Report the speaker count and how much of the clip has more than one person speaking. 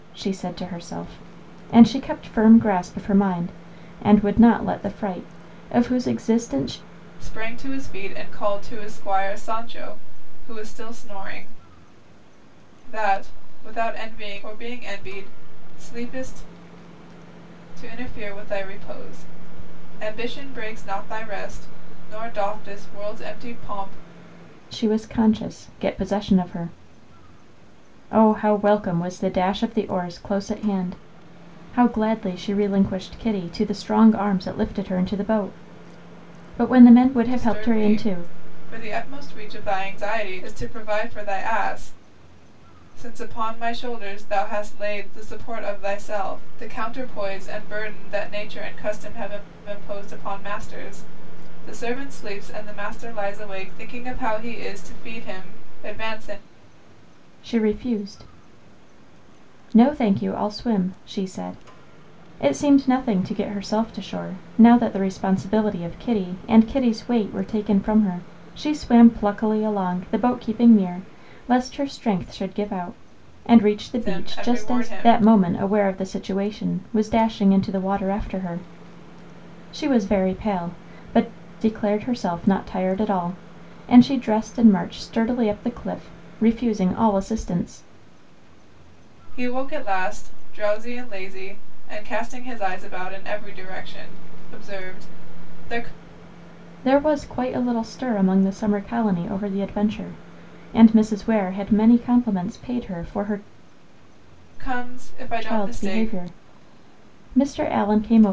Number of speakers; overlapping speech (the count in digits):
2, about 3%